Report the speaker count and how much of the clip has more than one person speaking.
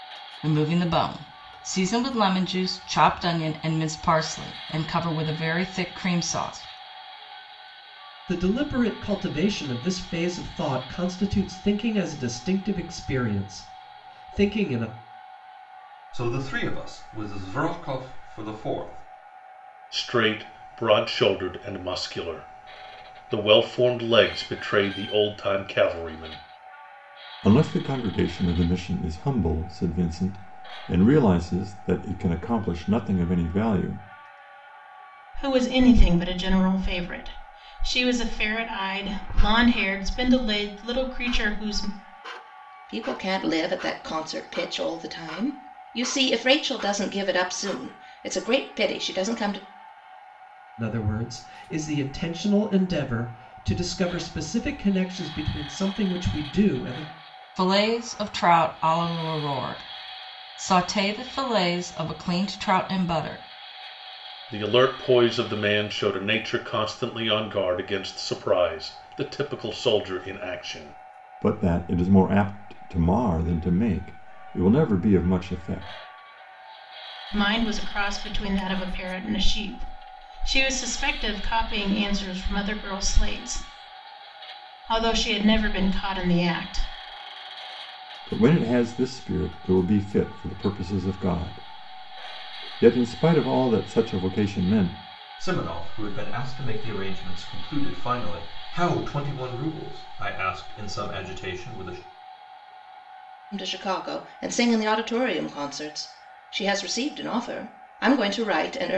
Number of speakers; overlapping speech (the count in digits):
7, no overlap